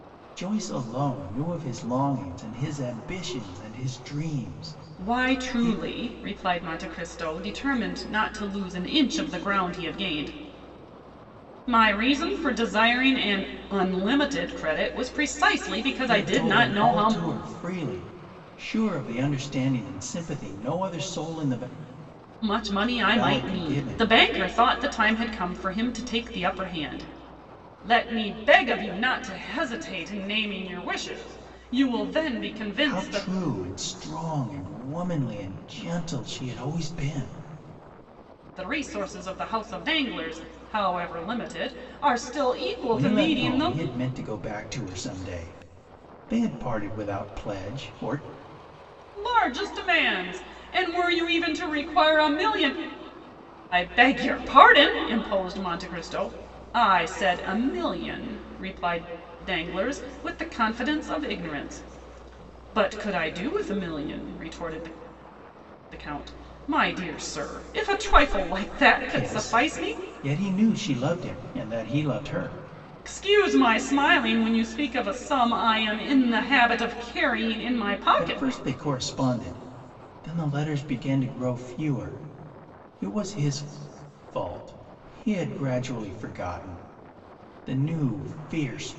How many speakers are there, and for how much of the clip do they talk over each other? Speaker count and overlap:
2, about 6%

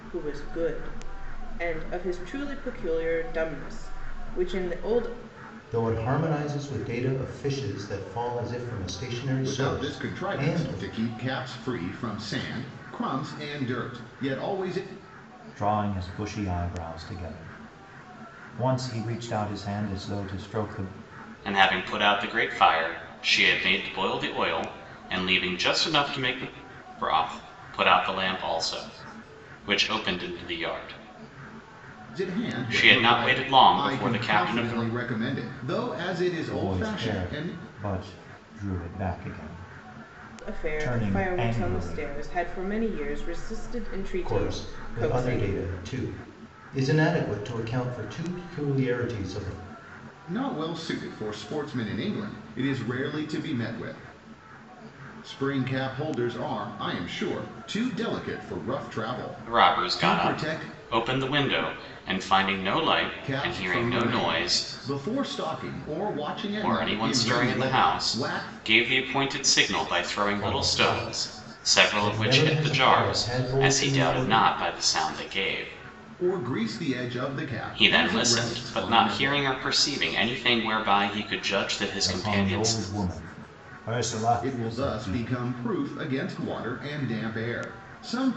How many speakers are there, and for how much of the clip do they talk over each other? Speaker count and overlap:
5, about 23%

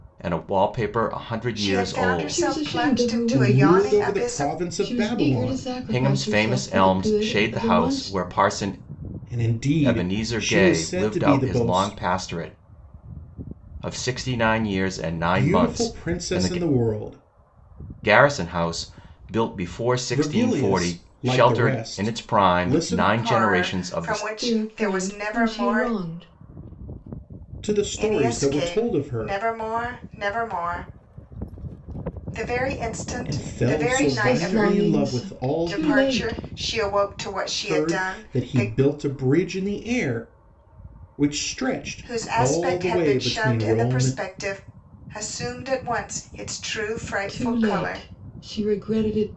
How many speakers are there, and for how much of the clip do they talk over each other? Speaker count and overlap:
4, about 49%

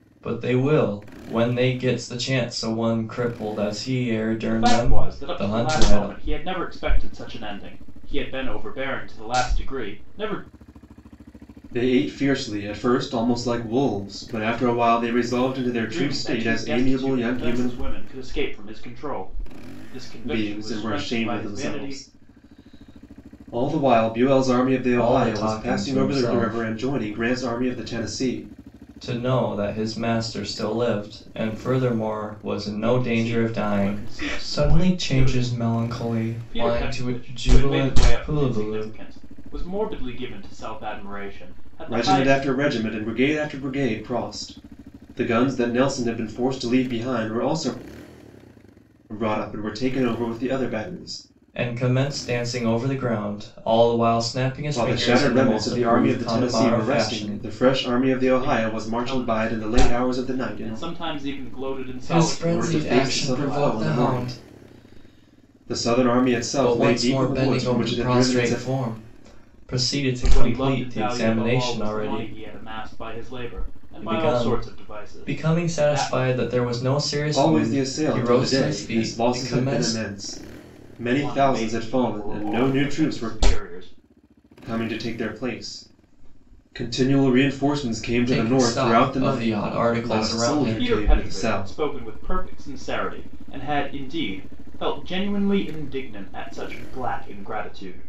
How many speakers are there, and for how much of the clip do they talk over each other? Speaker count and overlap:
3, about 36%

